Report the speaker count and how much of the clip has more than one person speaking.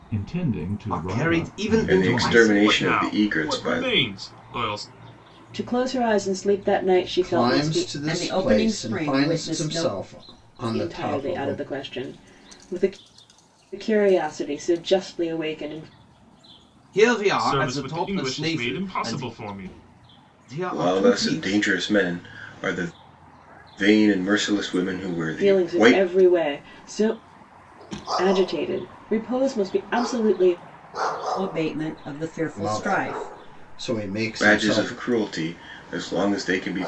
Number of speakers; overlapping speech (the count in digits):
7, about 31%